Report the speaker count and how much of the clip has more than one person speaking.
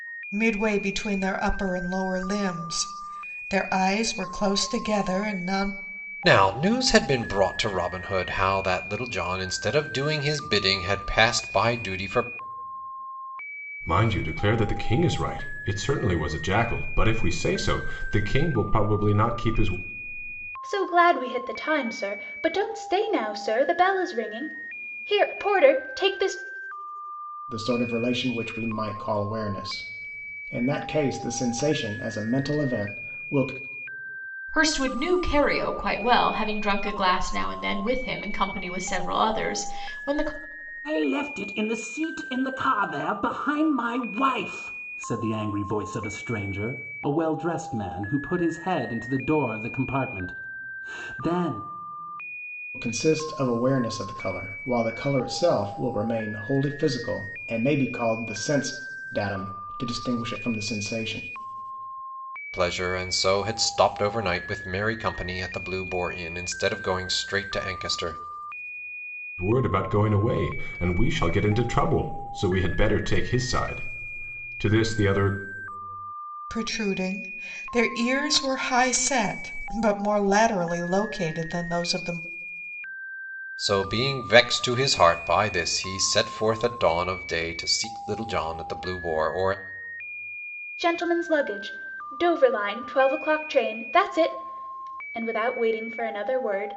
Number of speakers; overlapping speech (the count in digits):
7, no overlap